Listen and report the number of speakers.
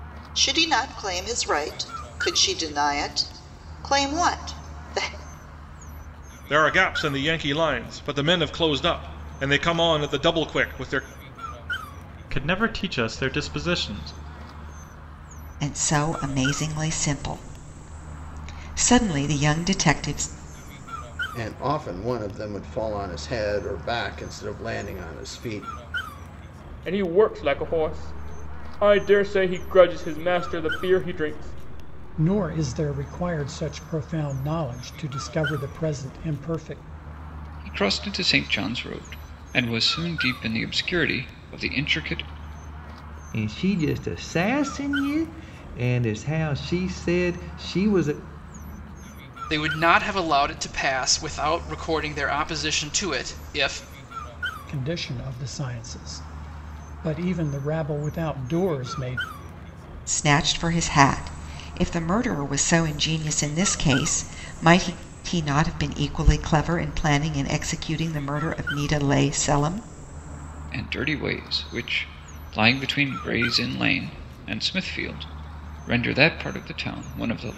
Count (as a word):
ten